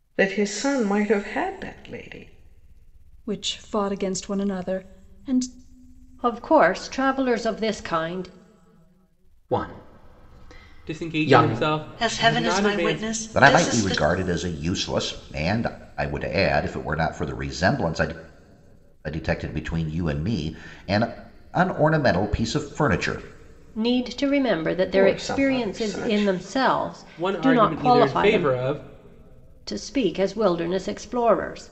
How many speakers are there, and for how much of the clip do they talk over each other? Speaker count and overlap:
7, about 17%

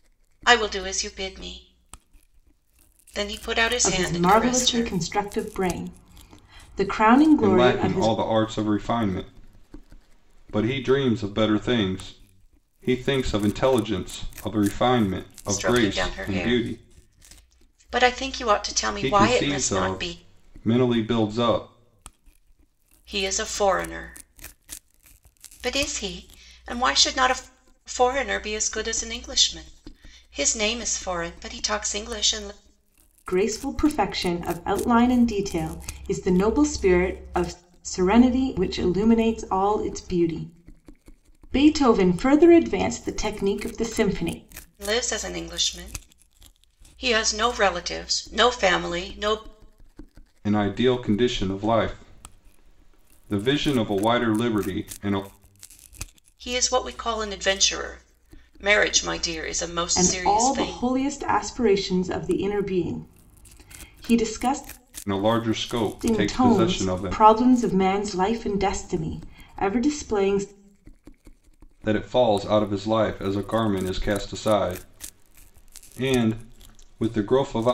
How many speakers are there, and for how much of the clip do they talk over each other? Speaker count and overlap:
3, about 9%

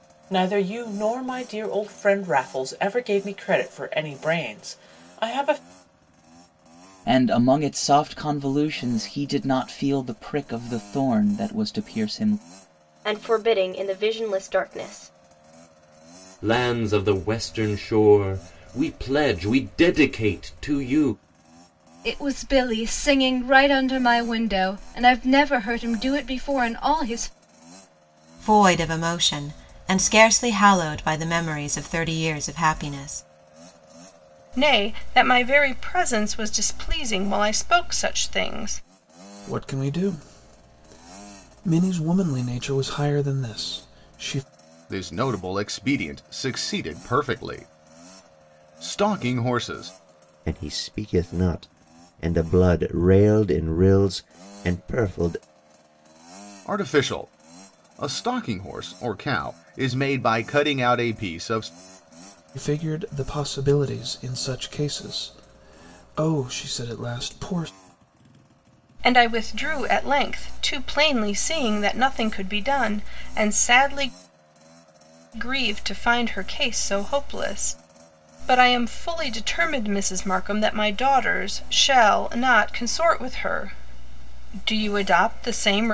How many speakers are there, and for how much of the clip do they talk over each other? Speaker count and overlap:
10, no overlap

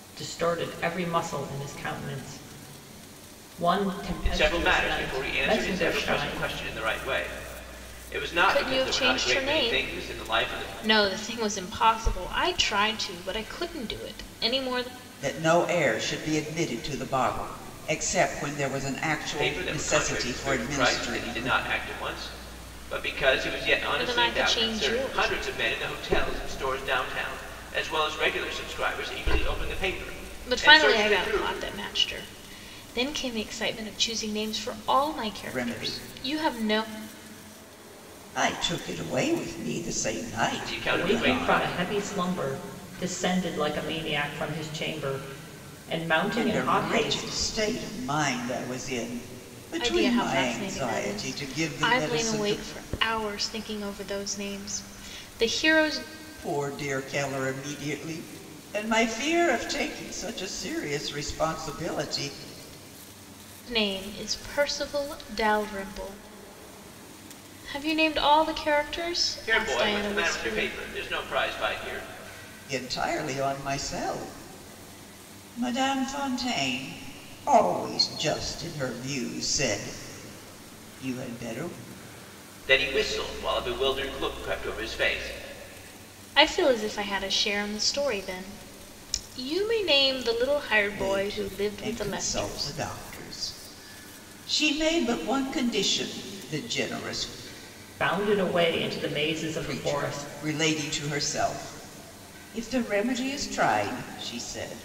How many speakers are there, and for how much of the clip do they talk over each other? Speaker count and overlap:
4, about 19%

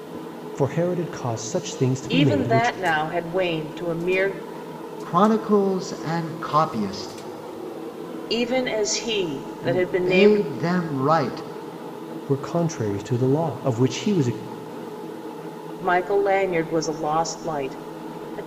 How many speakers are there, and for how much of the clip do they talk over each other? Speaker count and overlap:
3, about 9%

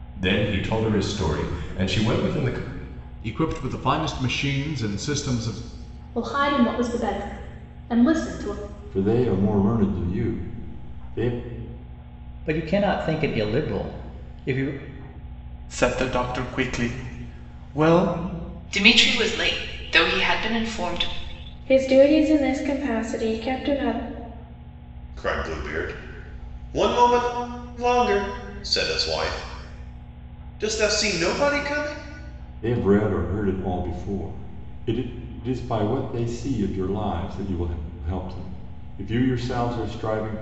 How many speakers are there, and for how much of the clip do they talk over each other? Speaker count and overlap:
9, no overlap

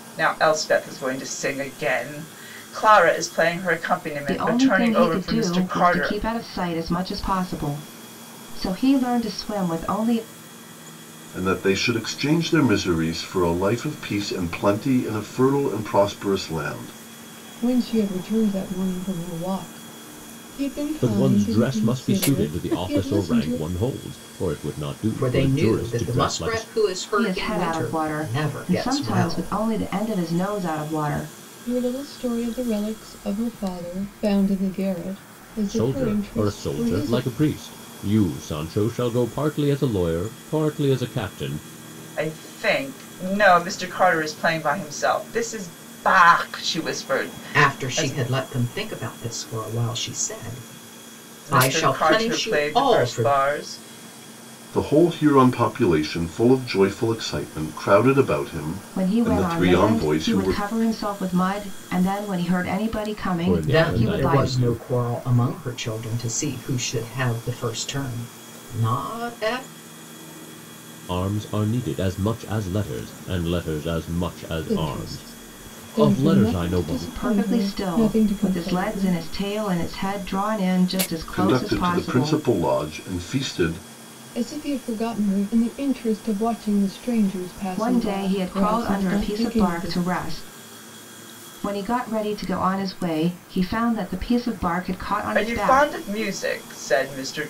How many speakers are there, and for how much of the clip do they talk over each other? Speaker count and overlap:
6, about 25%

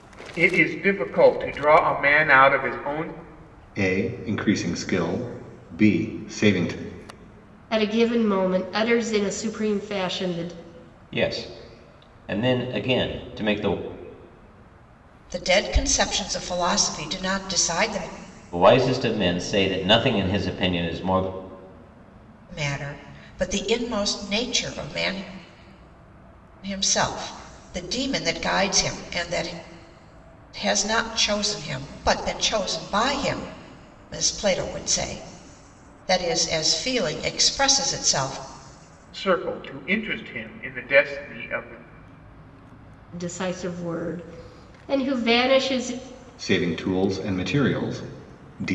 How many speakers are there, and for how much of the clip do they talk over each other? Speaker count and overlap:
5, no overlap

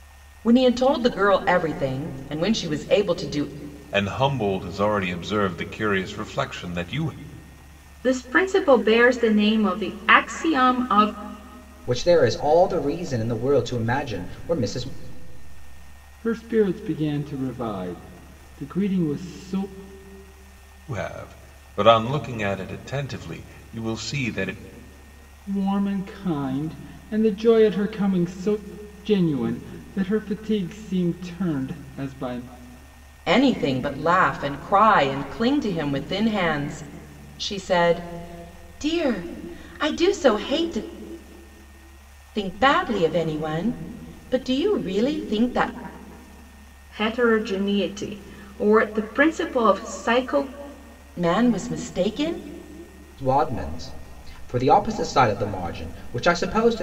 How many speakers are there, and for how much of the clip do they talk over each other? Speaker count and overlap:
5, no overlap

